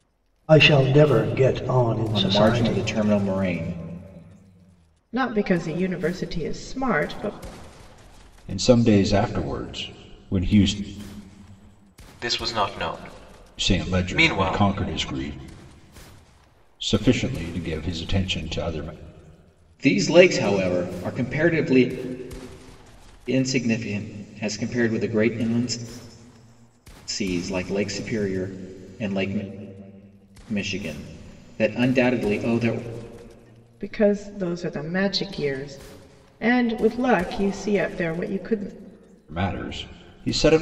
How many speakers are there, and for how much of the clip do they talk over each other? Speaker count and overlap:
5, about 5%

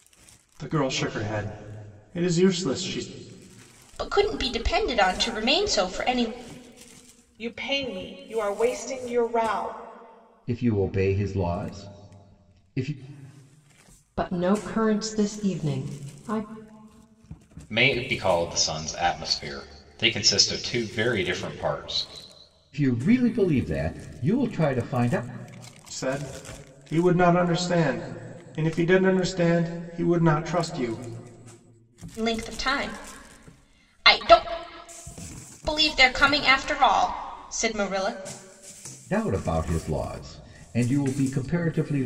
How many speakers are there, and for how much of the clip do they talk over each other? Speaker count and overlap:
6, no overlap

